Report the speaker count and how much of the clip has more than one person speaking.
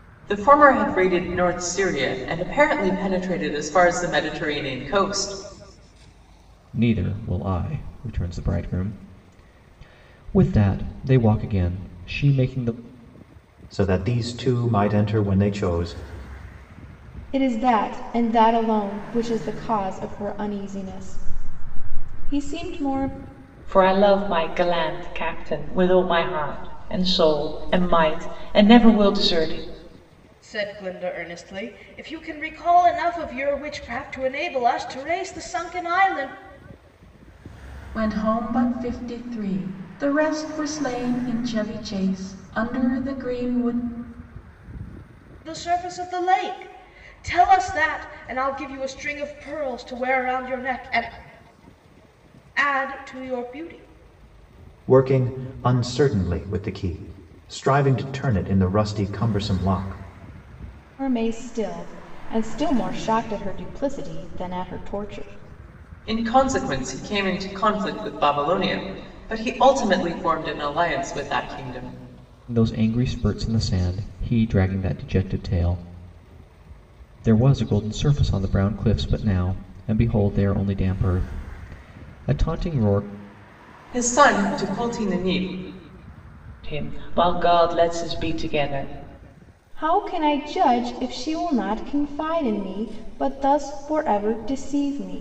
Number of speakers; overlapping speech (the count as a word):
seven, no overlap